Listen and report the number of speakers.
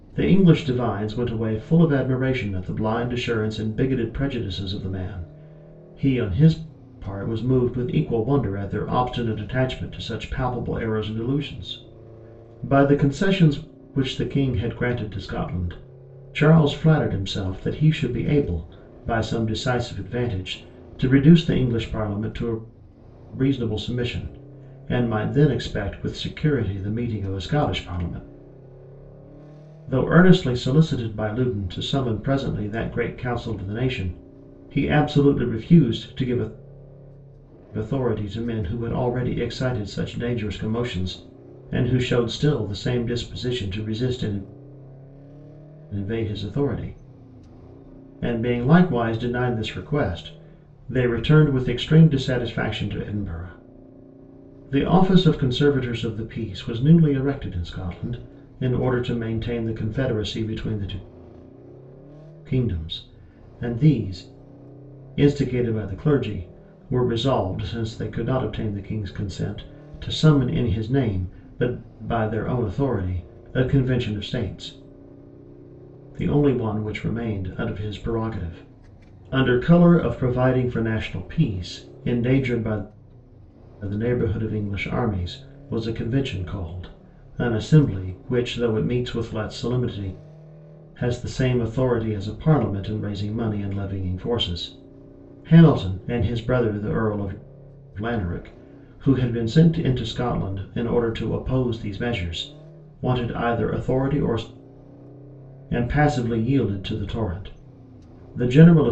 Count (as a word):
one